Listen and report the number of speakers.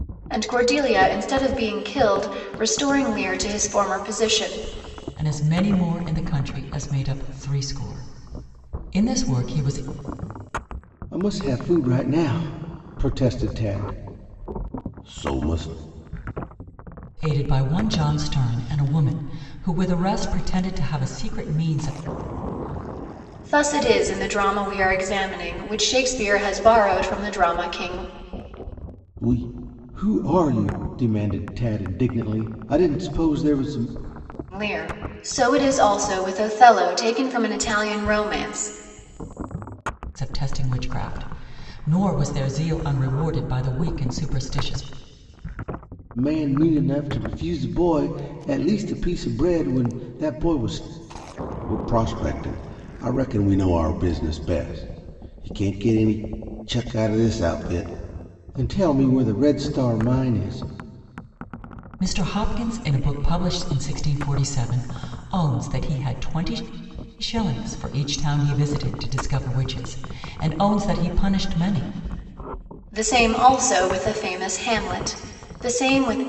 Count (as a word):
three